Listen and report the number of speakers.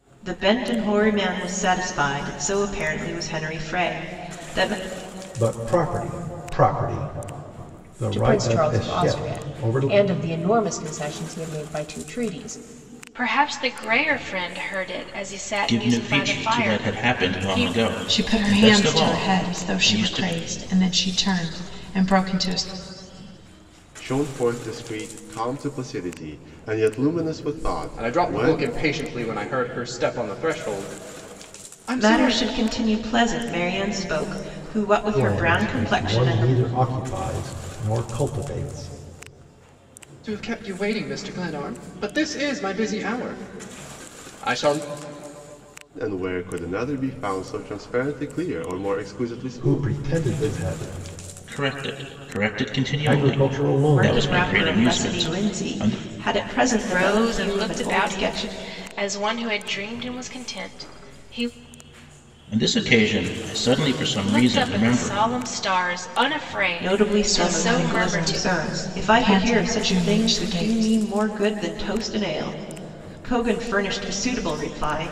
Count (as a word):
eight